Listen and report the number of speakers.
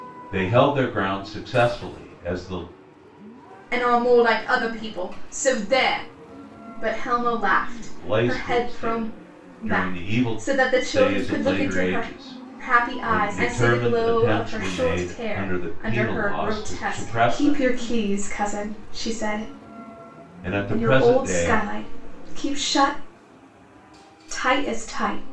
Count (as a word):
two